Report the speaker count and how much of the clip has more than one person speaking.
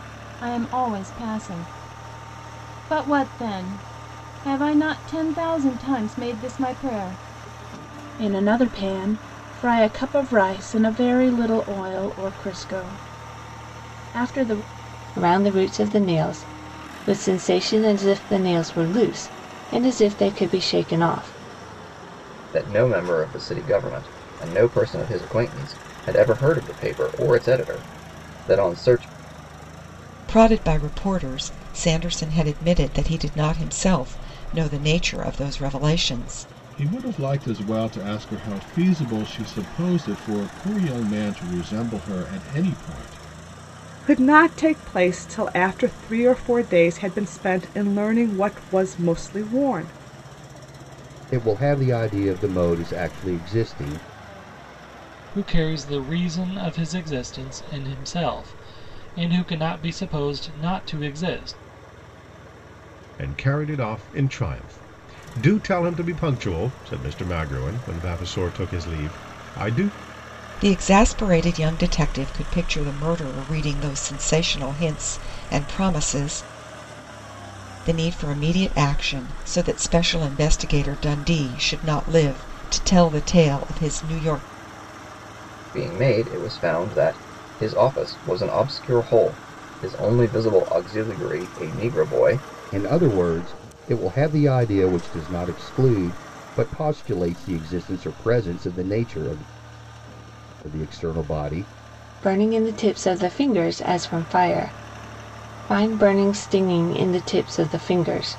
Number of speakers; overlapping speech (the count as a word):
ten, no overlap